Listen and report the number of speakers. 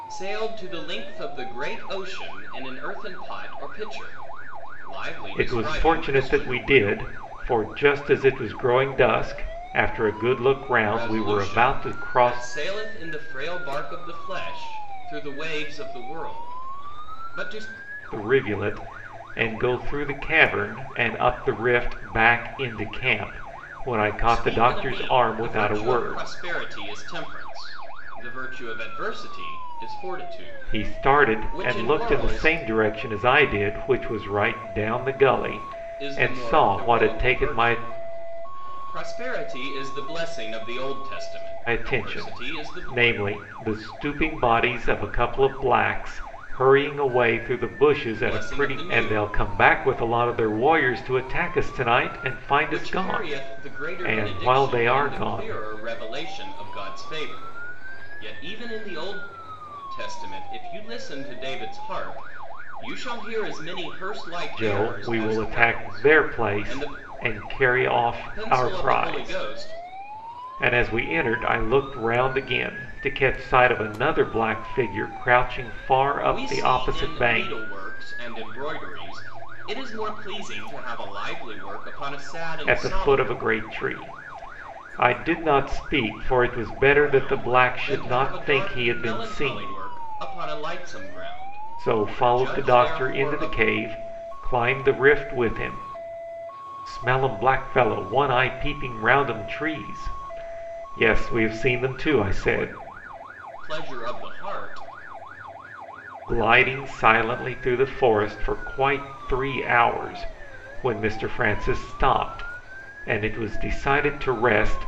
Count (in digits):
2